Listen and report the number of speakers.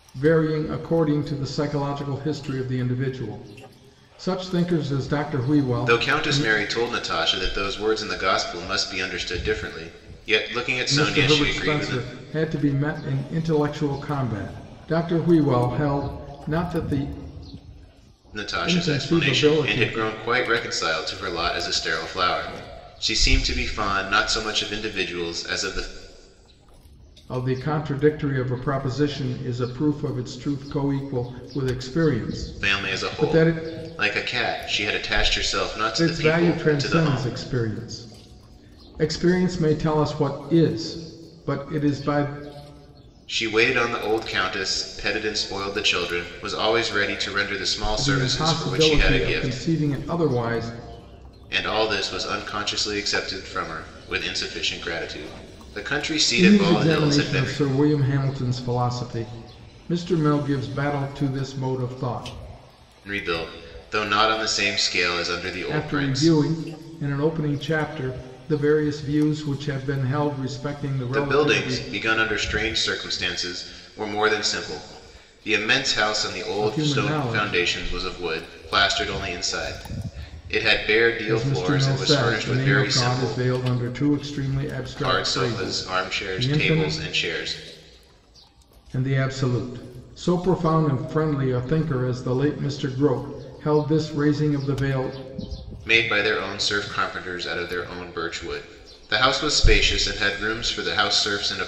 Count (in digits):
2